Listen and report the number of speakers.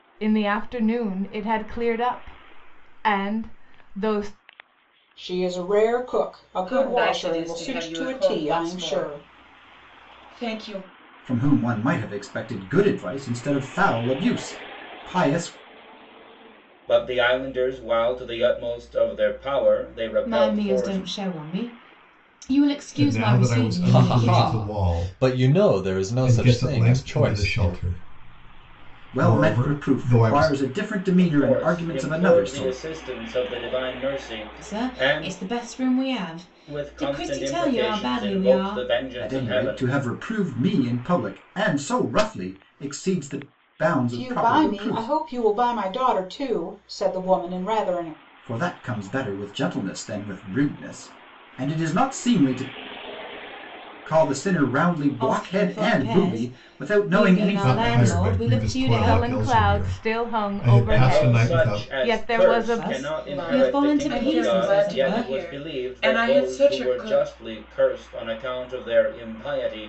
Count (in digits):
8